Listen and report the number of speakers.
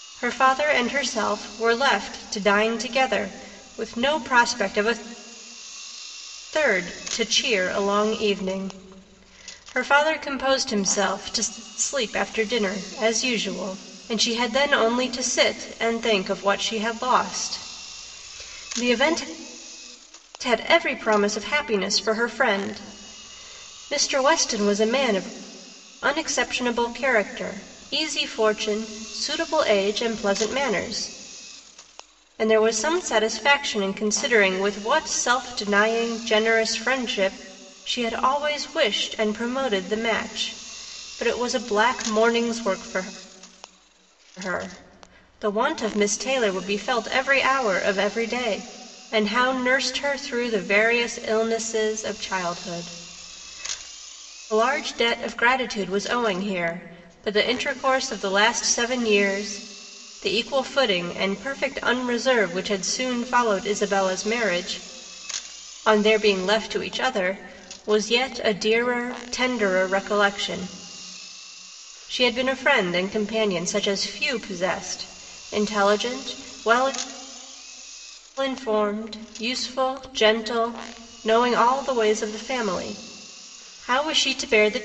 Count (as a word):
one